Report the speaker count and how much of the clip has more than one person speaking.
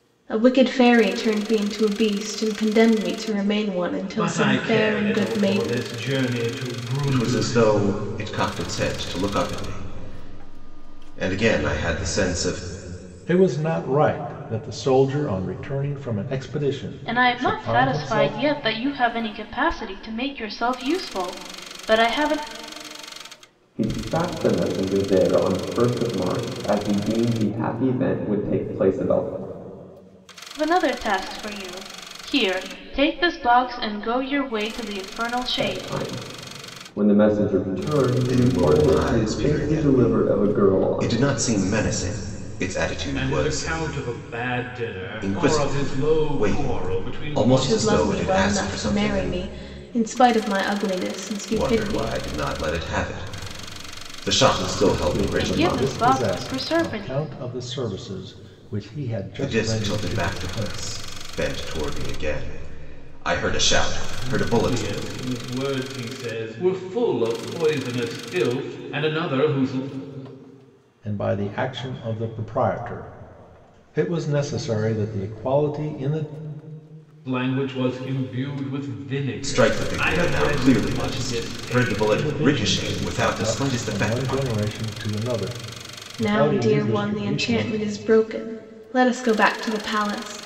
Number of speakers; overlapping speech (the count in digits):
6, about 27%